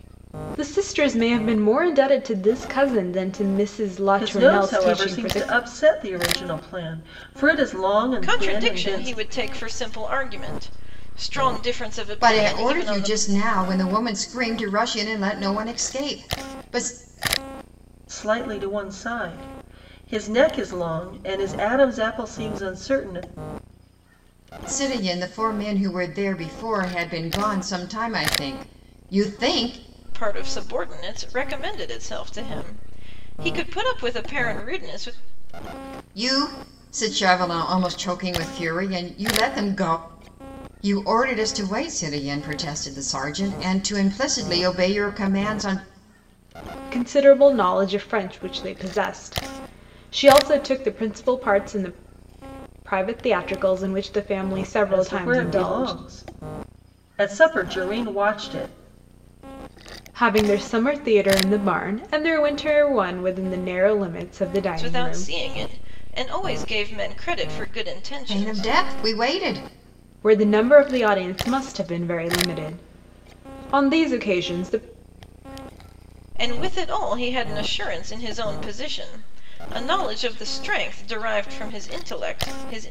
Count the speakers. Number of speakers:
four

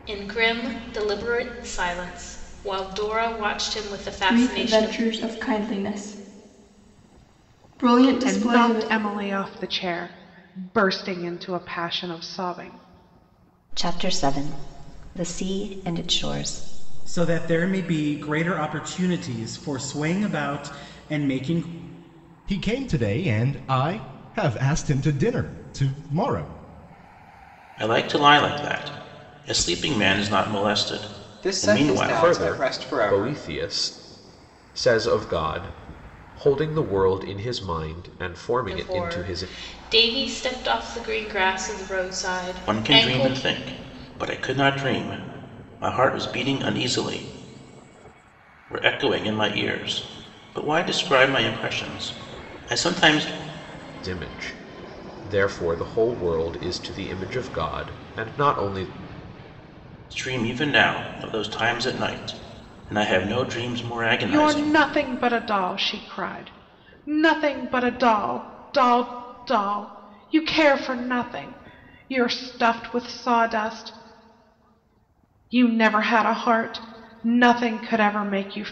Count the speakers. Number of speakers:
nine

